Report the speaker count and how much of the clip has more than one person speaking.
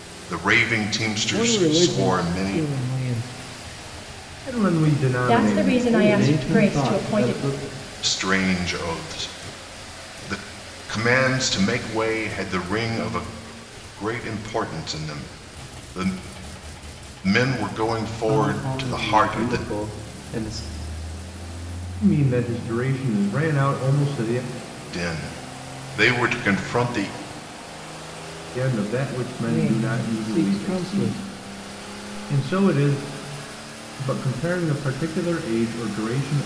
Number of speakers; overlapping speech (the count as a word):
five, about 19%